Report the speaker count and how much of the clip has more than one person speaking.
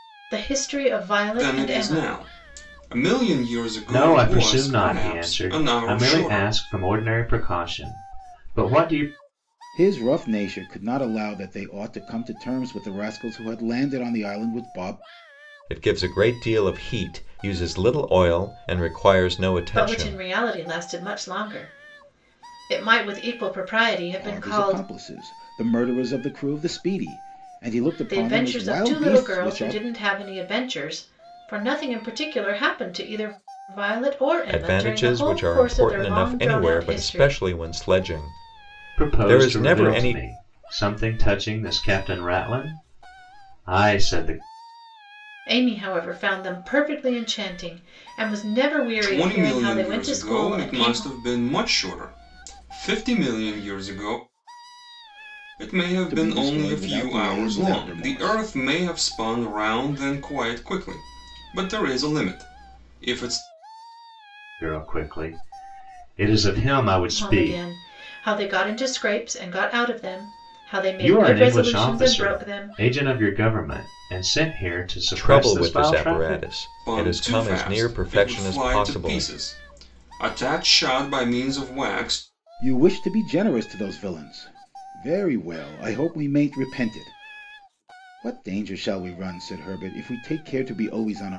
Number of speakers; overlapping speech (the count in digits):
5, about 24%